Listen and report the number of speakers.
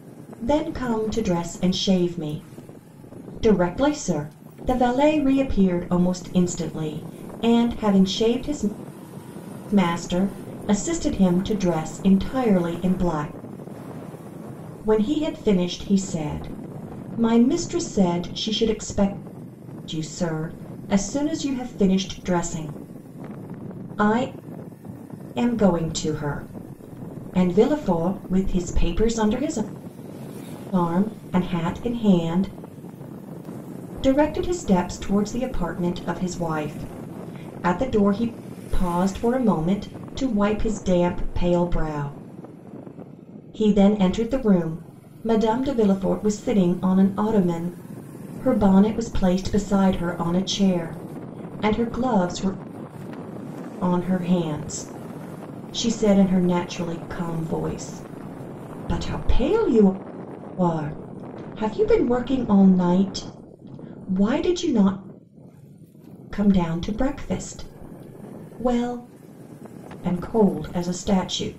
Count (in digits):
1